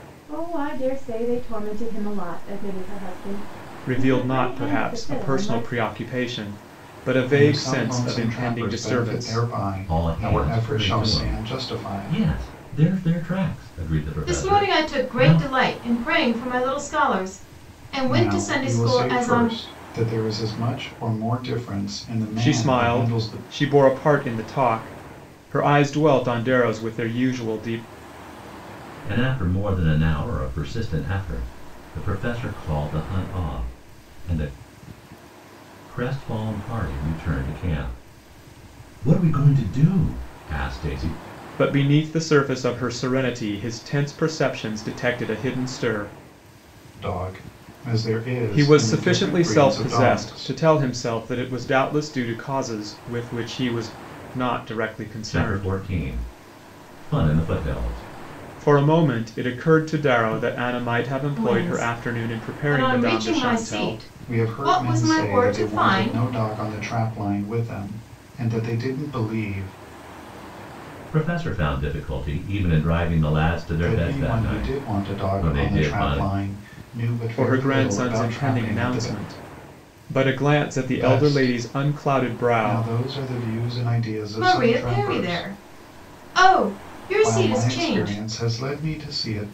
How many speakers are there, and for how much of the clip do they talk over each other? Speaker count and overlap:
5, about 32%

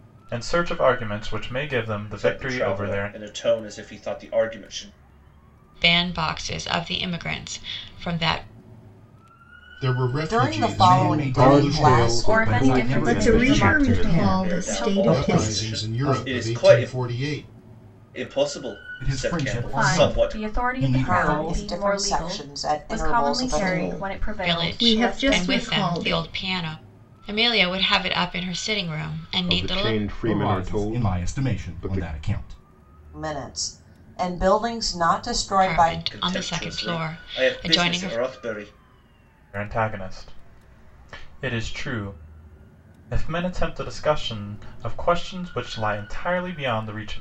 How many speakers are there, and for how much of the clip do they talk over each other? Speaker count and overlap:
10, about 42%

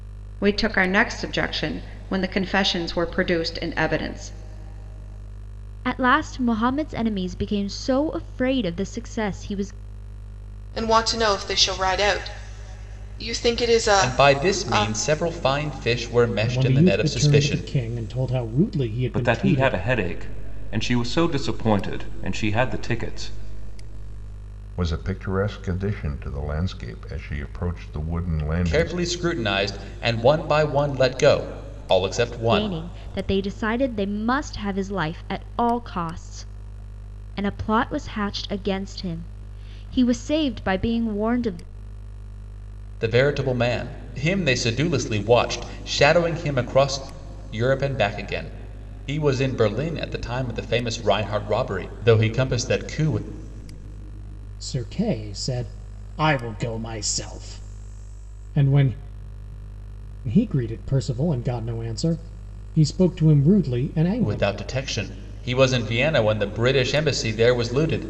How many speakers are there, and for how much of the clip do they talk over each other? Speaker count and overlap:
7, about 6%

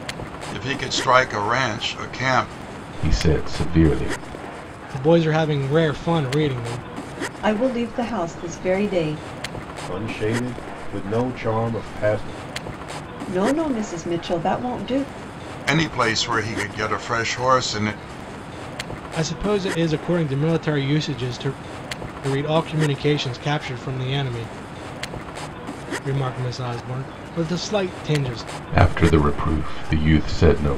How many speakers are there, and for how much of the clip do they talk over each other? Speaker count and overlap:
5, no overlap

